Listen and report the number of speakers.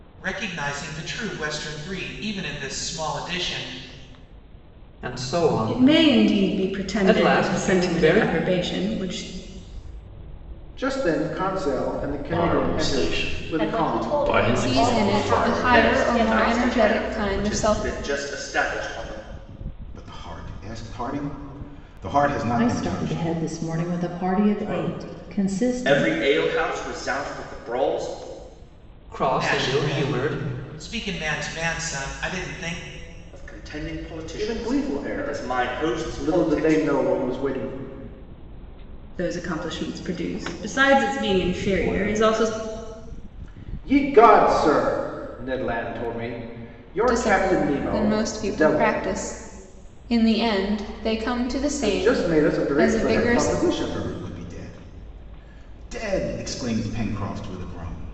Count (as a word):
ten